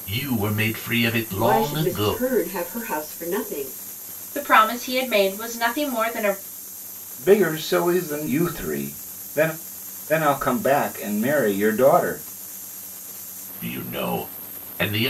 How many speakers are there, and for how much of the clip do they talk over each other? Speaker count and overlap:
four, about 6%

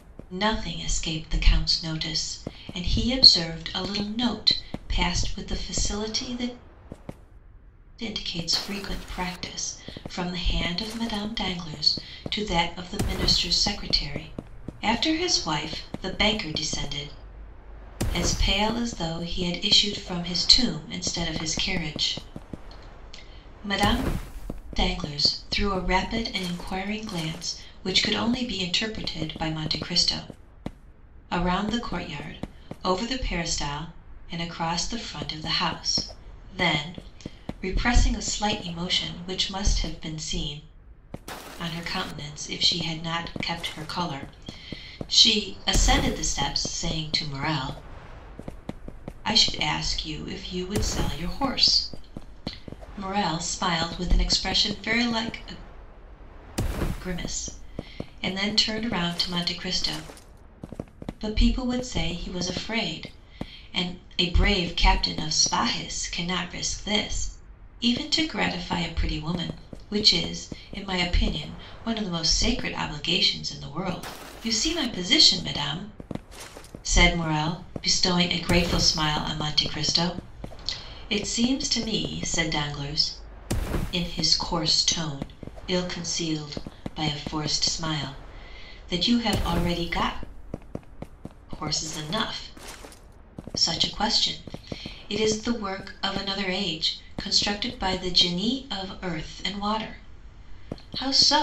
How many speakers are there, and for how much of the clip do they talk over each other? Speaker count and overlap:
one, no overlap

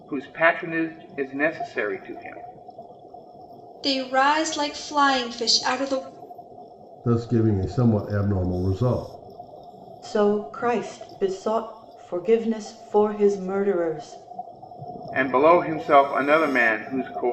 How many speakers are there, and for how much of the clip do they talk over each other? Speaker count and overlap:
four, no overlap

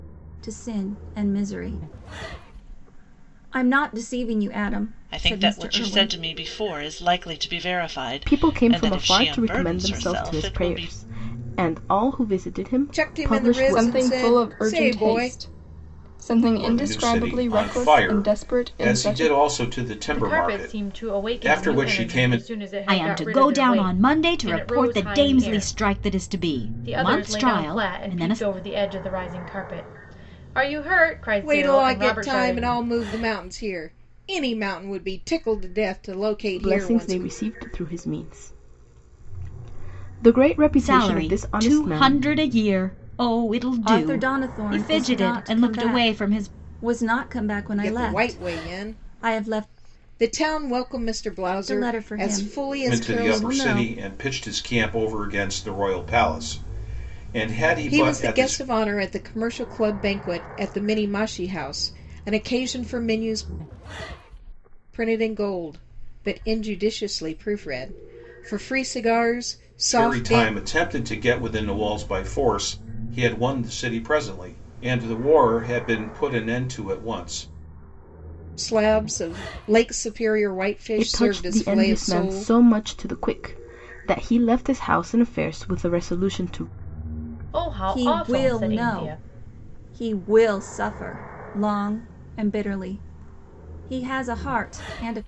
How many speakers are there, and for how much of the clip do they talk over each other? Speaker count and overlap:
eight, about 32%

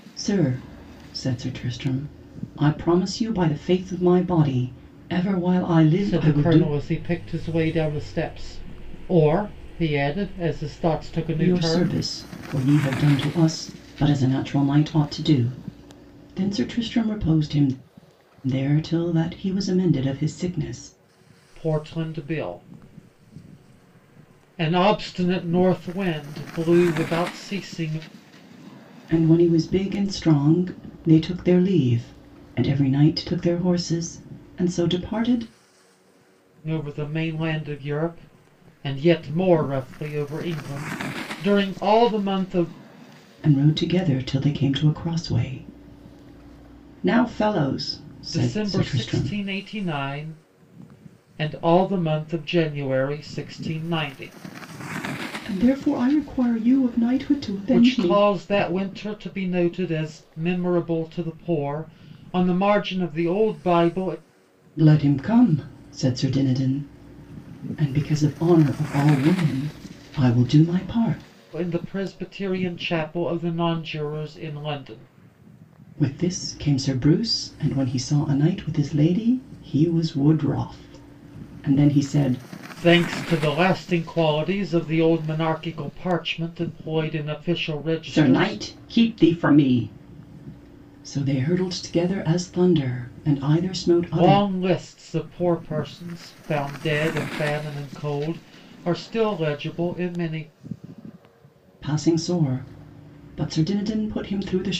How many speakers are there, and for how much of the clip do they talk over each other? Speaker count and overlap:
two, about 4%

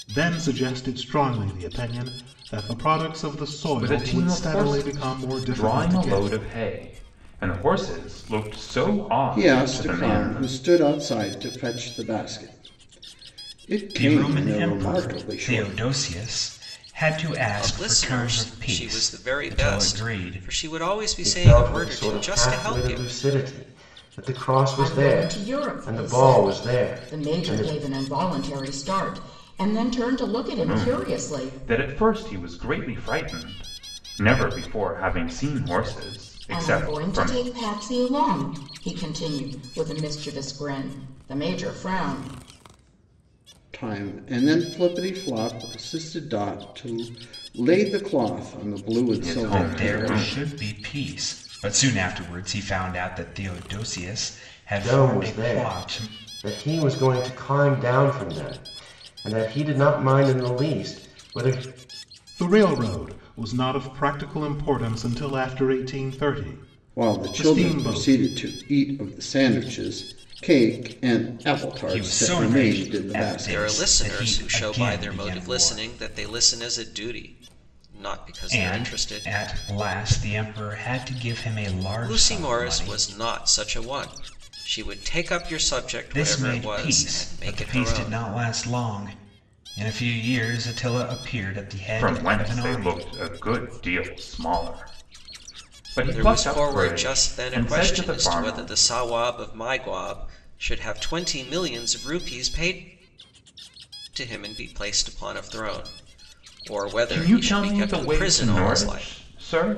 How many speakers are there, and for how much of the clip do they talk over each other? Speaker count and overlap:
seven, about 30%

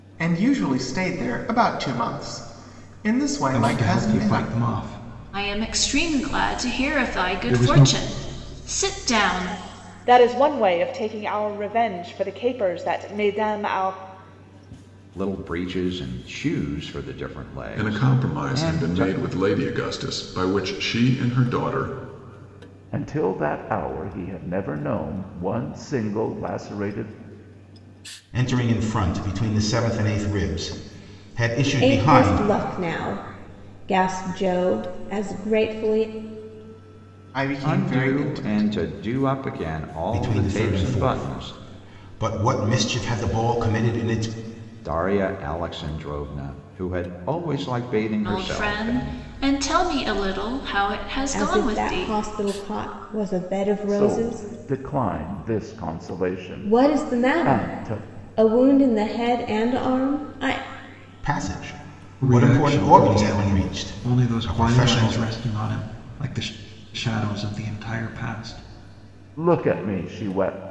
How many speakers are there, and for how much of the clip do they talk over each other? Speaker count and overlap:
nine, about 21%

